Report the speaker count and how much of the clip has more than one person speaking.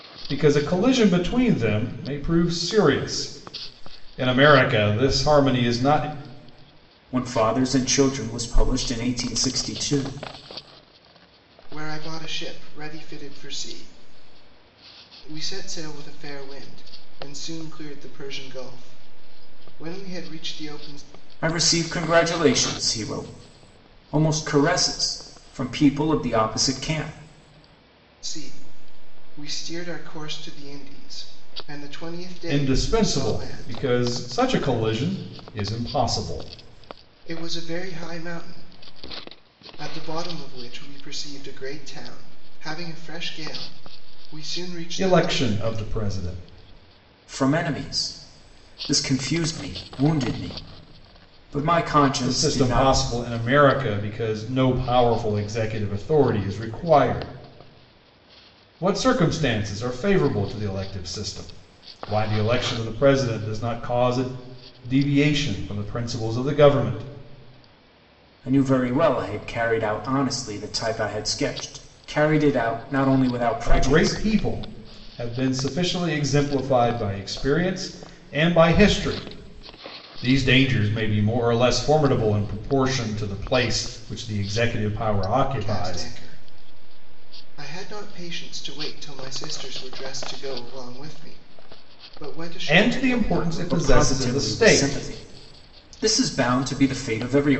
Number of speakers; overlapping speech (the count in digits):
3, about 7%